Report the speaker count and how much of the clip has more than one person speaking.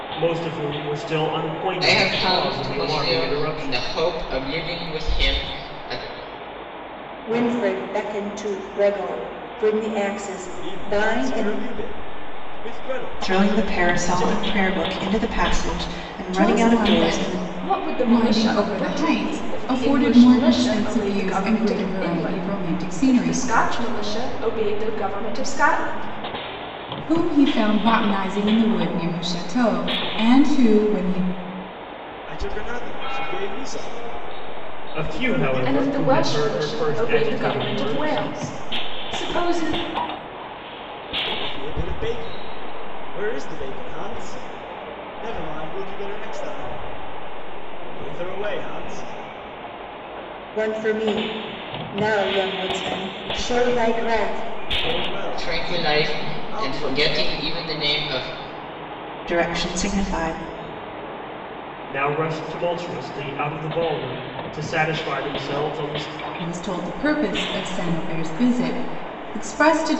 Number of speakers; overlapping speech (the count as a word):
seven, about 26%